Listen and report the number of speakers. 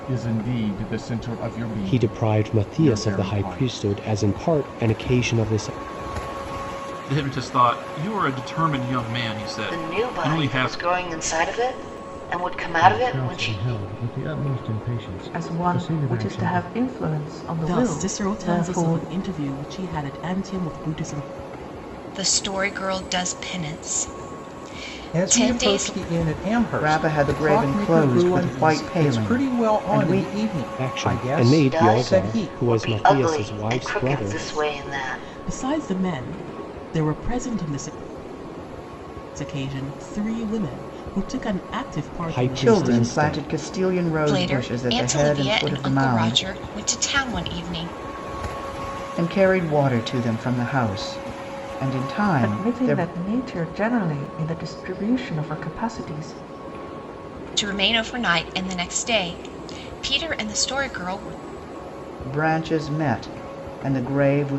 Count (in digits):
10